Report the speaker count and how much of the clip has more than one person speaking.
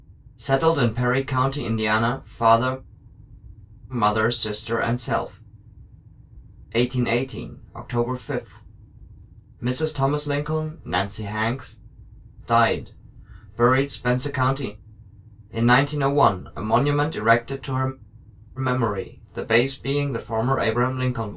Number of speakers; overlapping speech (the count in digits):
1, no overlap